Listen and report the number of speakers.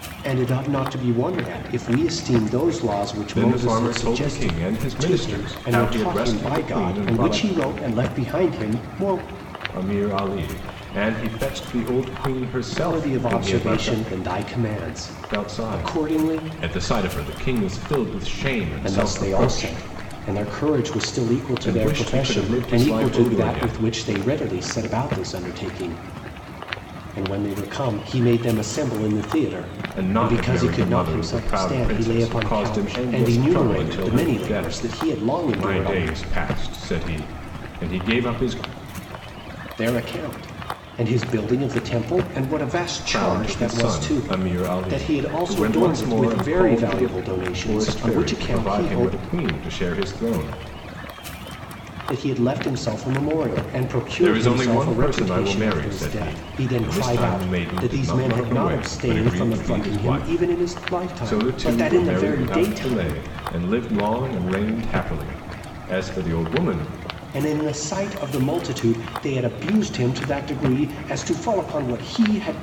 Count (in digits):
2